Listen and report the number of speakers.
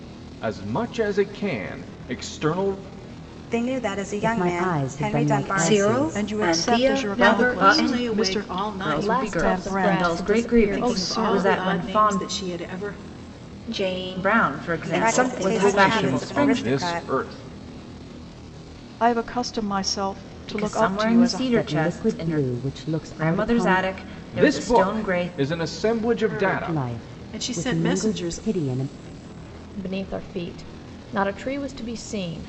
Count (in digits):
8